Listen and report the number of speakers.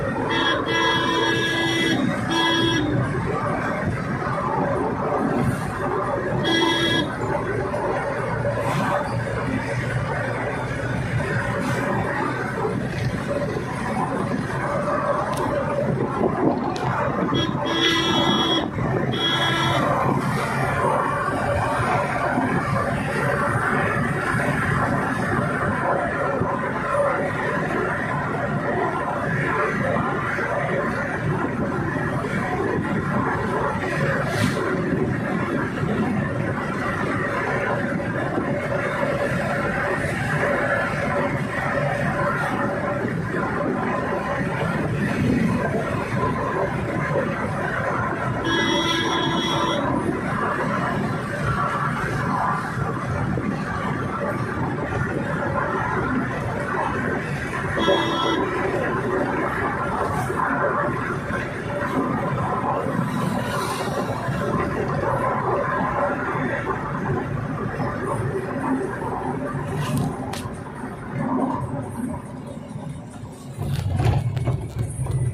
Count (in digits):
0